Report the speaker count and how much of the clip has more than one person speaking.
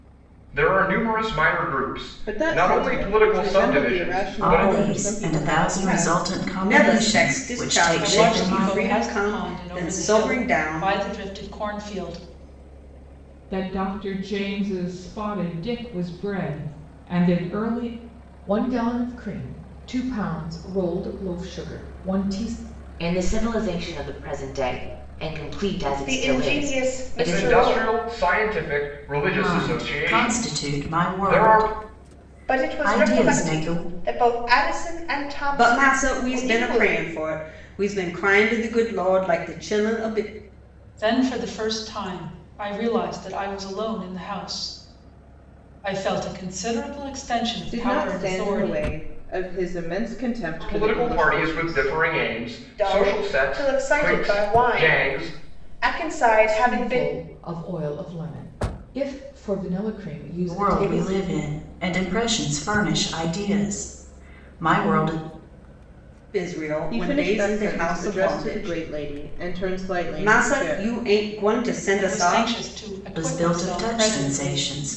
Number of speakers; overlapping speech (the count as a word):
nine, about 36%